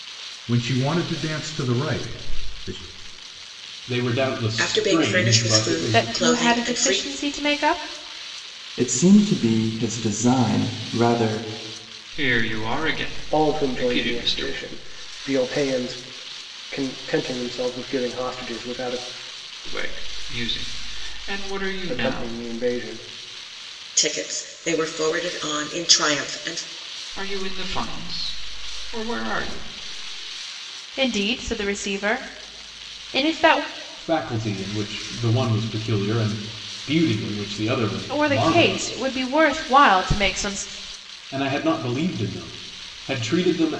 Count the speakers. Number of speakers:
7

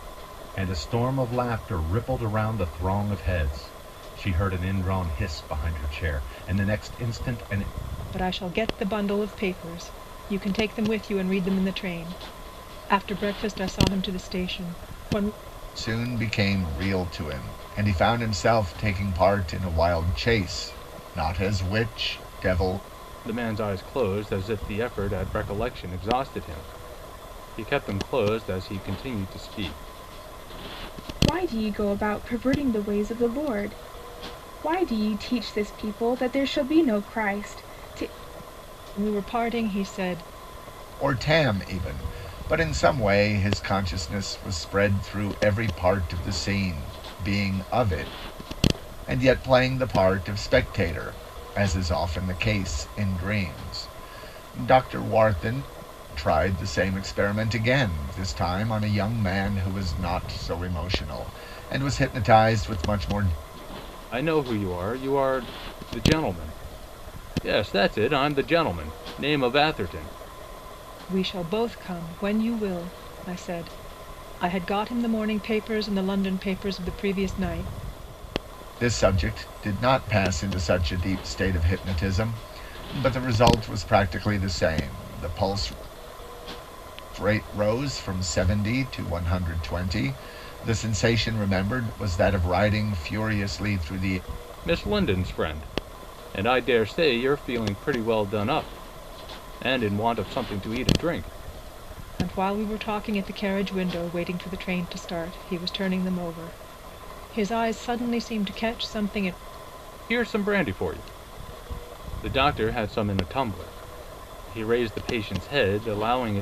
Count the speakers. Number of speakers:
5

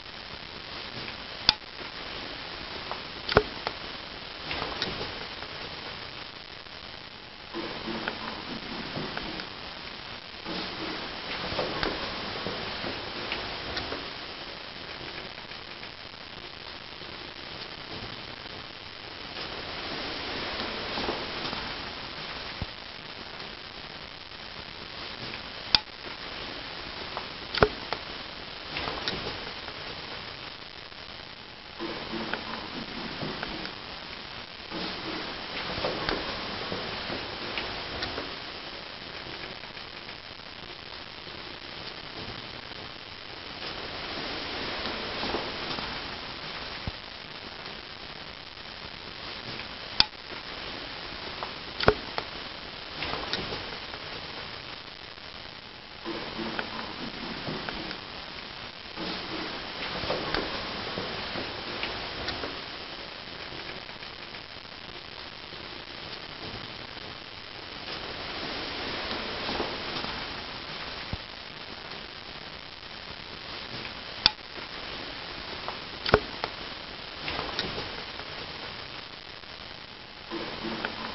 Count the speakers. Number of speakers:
0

